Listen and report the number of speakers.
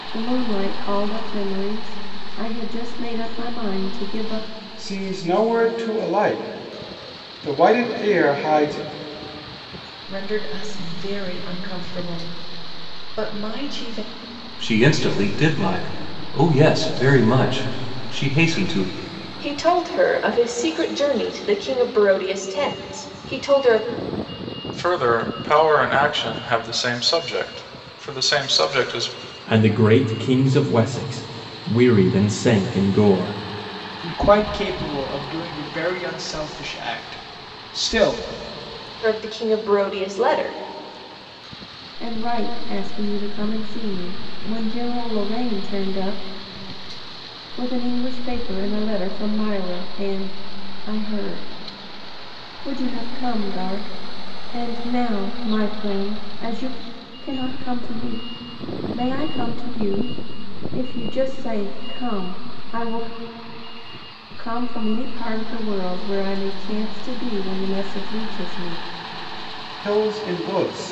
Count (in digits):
8